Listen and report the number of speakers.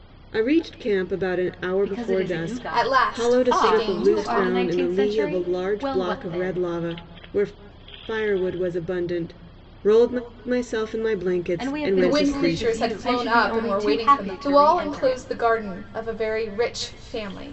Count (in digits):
3